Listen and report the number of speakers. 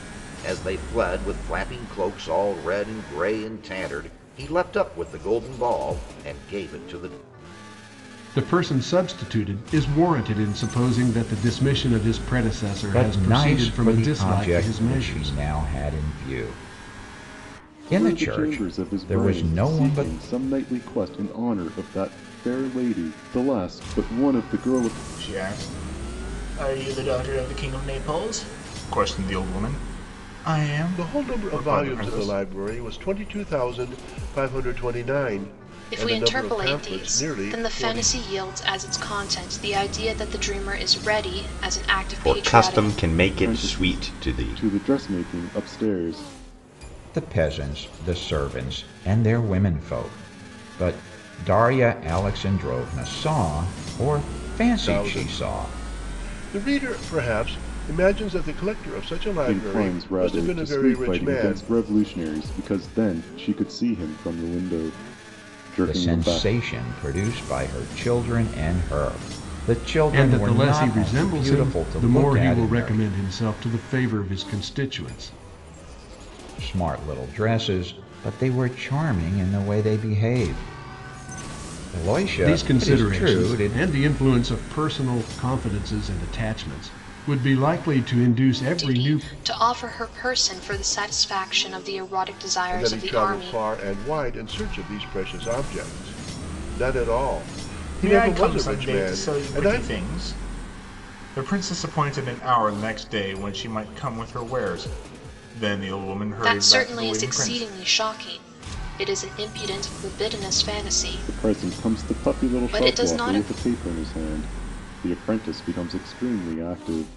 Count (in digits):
8